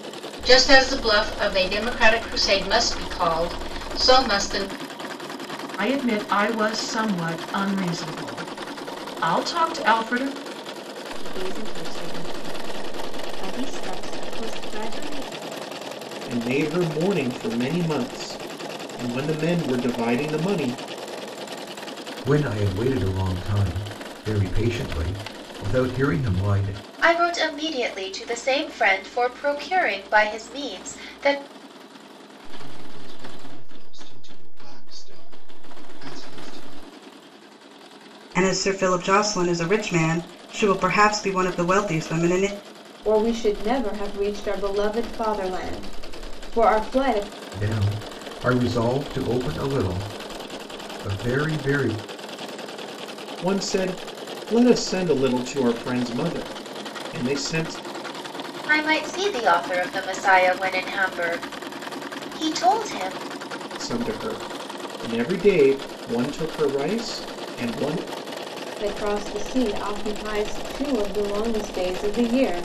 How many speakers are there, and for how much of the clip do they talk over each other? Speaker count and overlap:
nine, no overlap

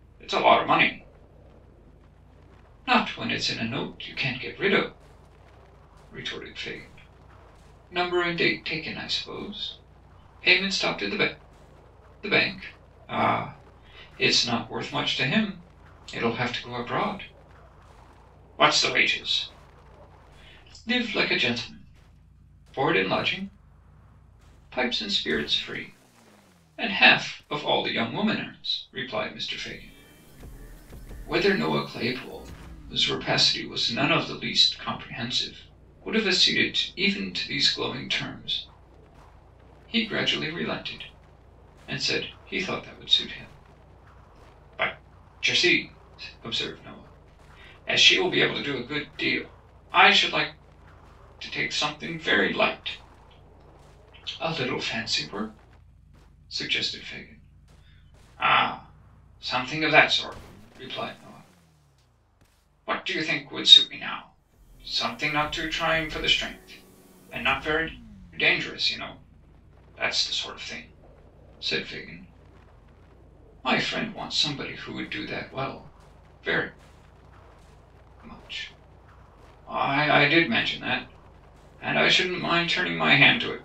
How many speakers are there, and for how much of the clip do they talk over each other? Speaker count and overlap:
one, no overlap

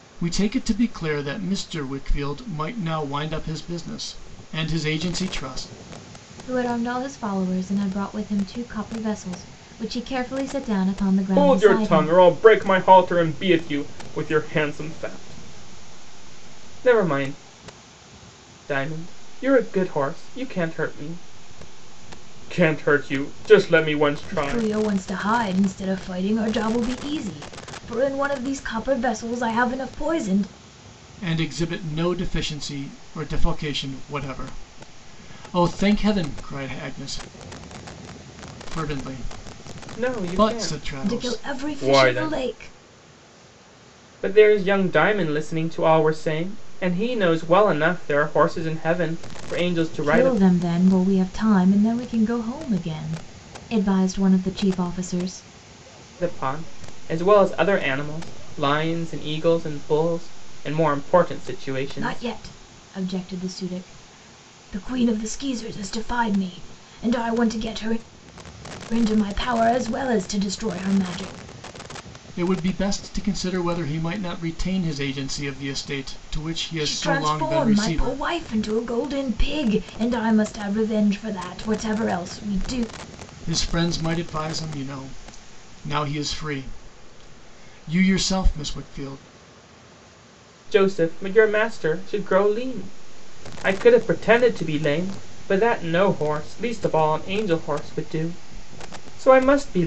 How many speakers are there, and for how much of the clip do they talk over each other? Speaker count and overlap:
three, about 6%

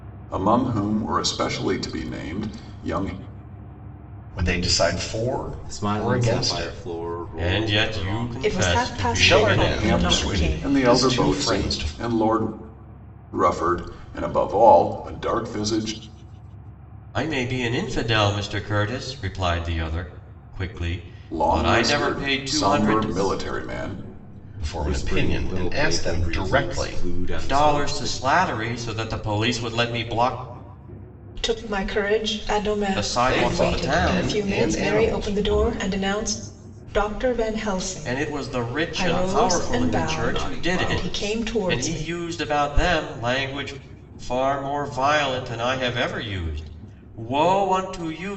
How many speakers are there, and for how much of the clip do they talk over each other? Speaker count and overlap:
five, about 39%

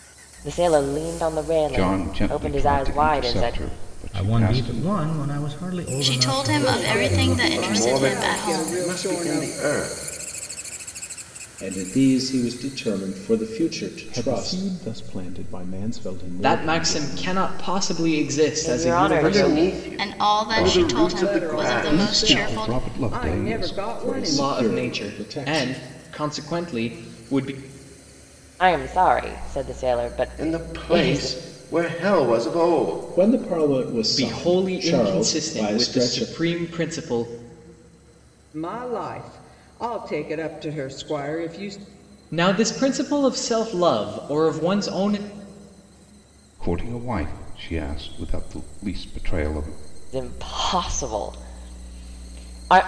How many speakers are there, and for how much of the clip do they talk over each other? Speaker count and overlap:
nine, about 35%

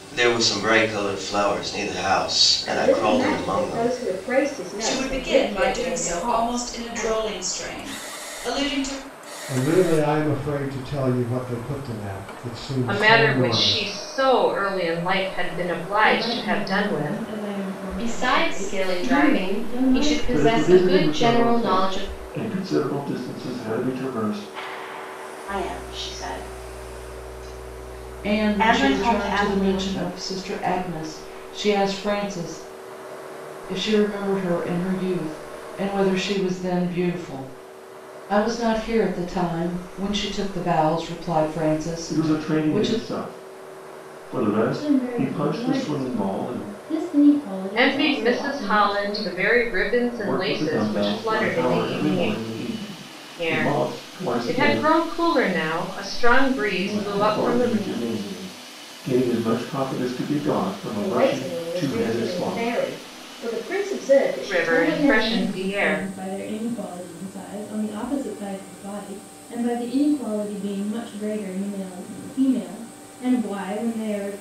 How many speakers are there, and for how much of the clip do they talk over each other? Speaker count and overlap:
ten, about 34%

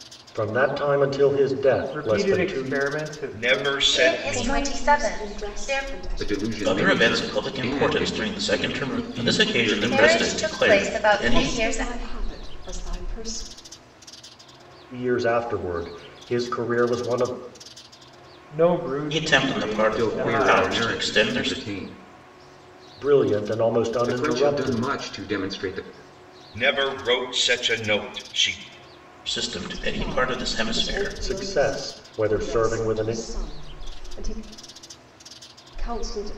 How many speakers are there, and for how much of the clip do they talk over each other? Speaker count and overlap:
seven, about 42%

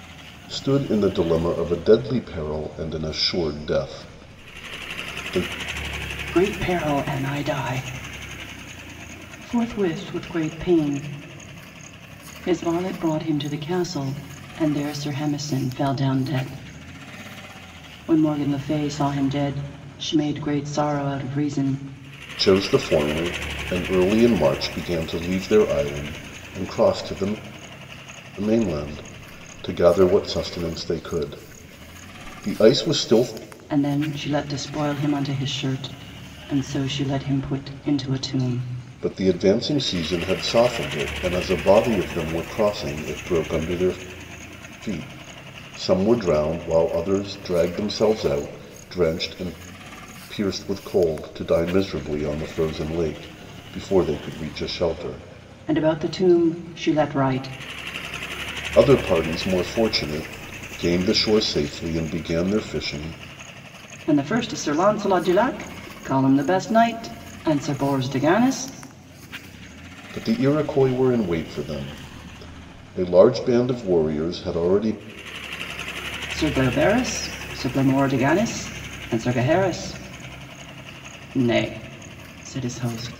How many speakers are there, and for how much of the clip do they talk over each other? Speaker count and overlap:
two, no overlap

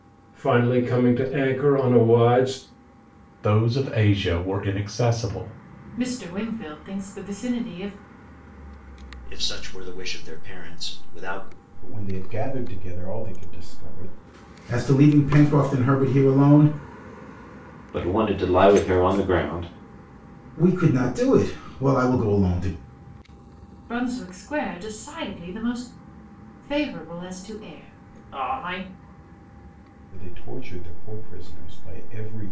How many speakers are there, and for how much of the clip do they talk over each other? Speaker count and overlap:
seven, no overlap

